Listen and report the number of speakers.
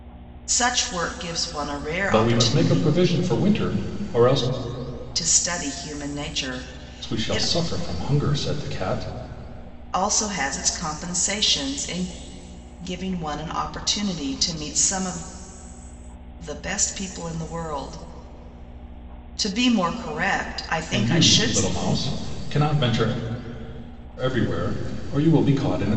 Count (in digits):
2